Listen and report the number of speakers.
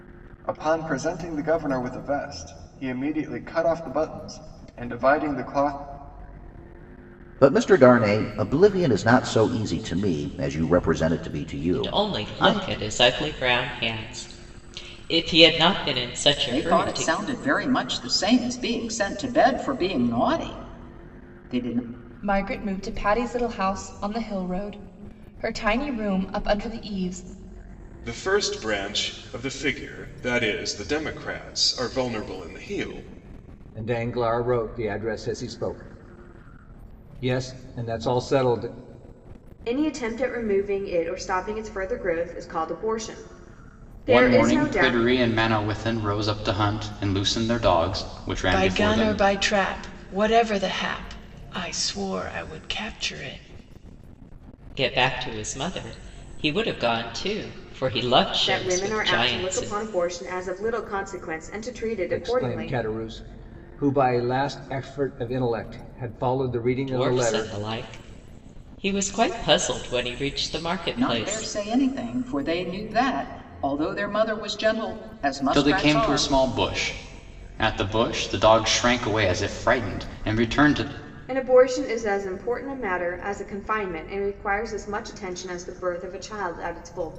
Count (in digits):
10